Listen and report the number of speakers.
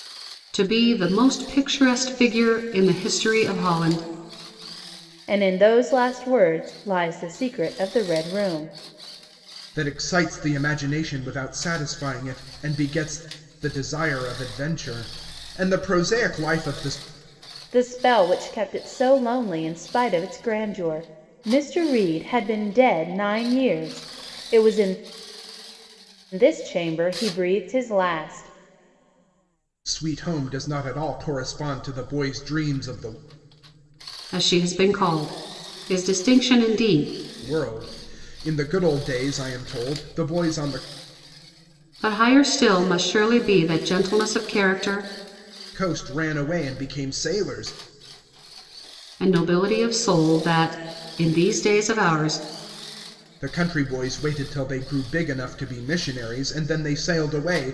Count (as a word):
three